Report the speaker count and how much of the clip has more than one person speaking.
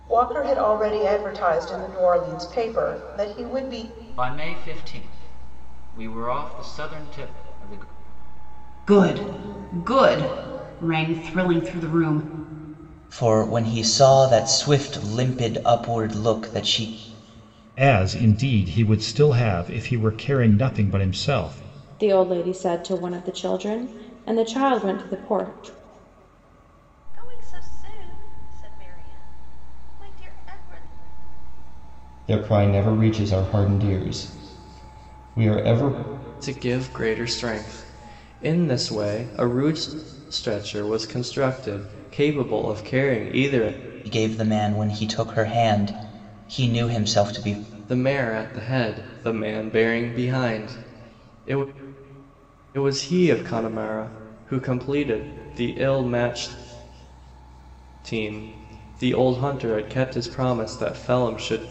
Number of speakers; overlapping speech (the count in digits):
9, no overlap